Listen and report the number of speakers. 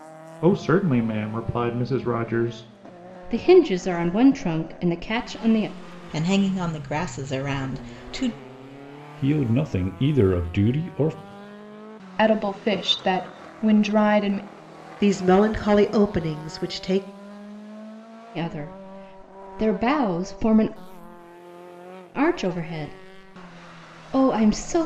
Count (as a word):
six